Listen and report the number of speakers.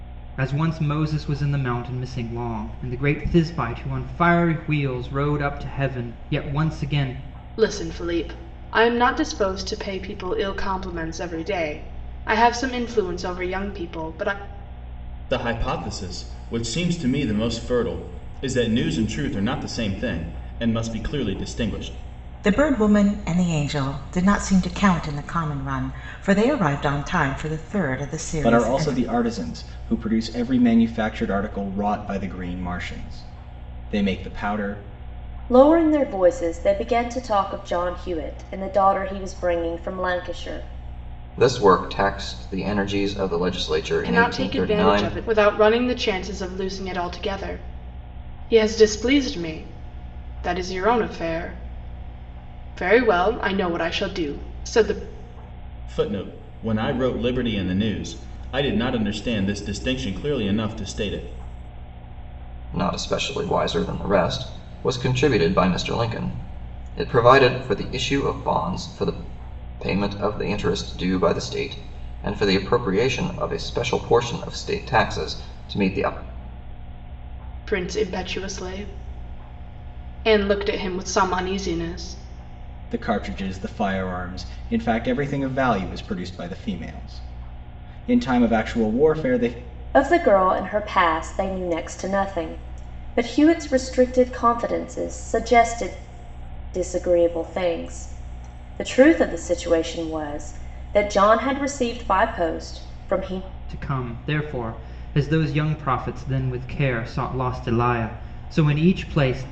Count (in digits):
7